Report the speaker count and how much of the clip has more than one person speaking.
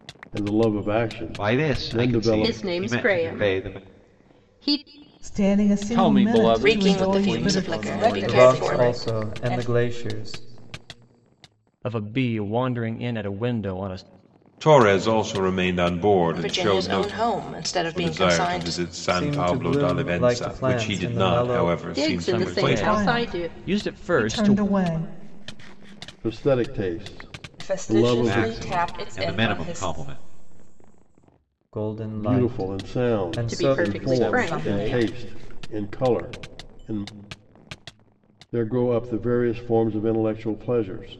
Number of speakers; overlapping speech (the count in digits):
10, about 45%